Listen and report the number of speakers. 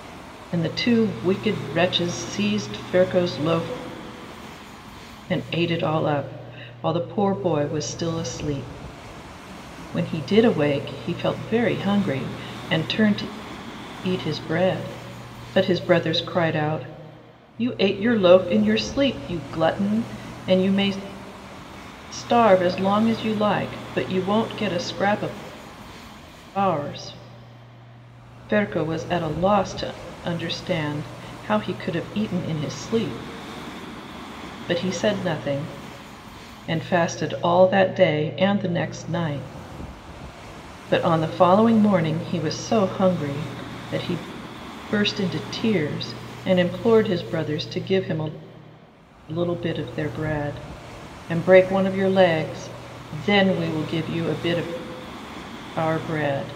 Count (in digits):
1